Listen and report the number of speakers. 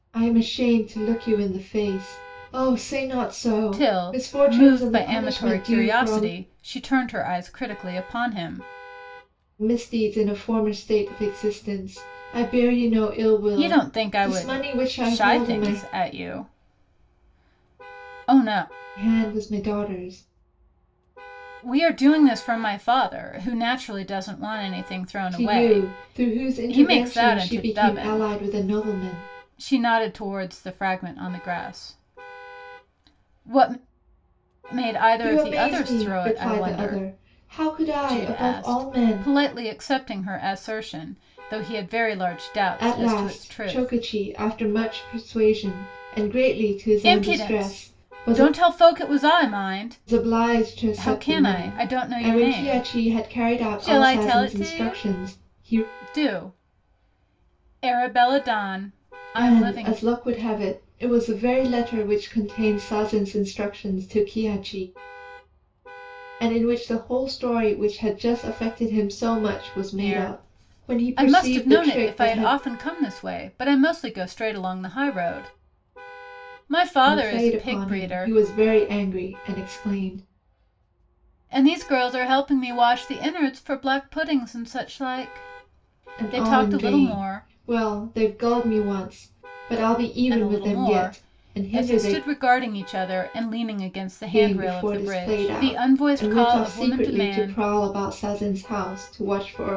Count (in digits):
2